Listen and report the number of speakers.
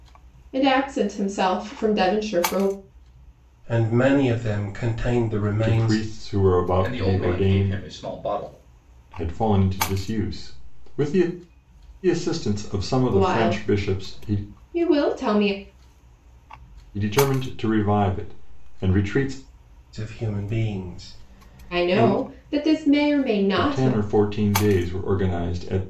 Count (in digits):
4